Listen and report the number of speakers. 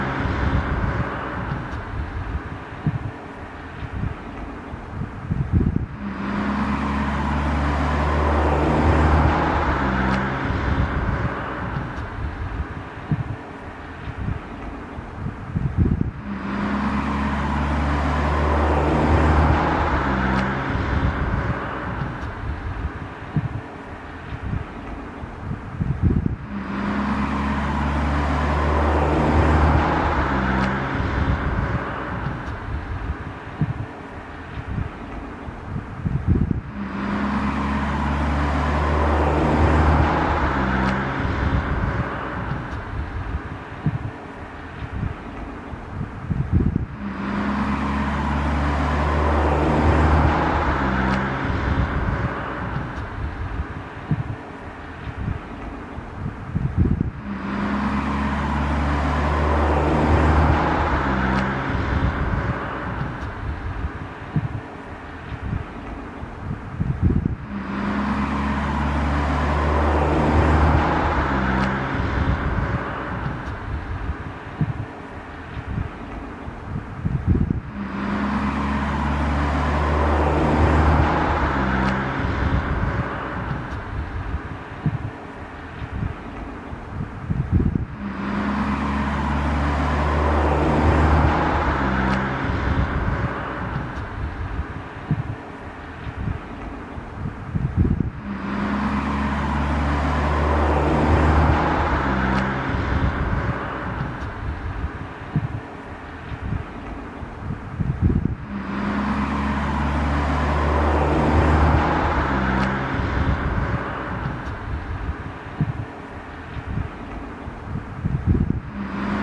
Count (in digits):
0